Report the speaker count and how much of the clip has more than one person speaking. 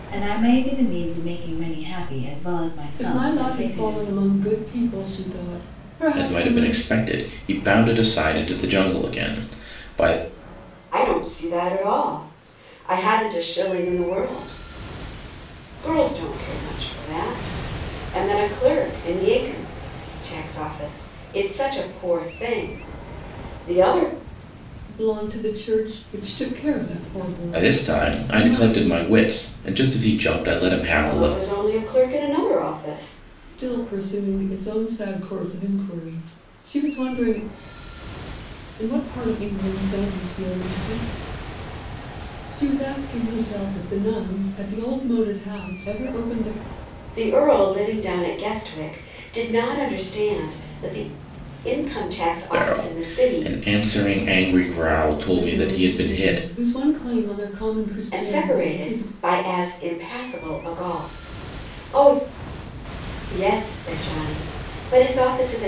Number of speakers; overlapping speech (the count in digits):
4, about 11%